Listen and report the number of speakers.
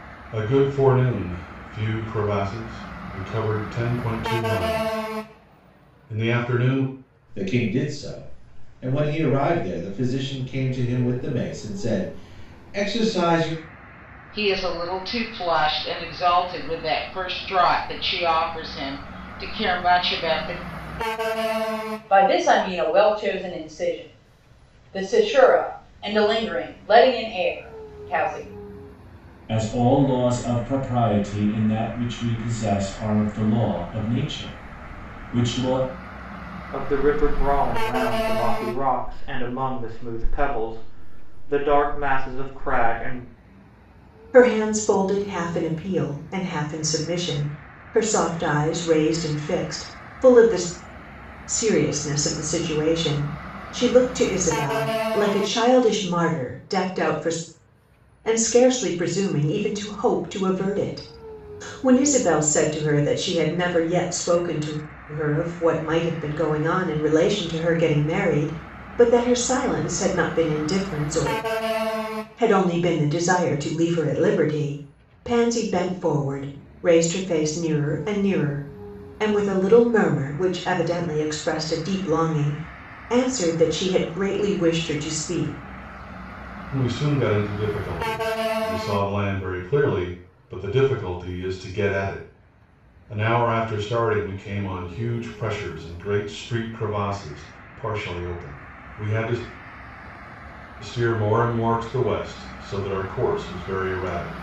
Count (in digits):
7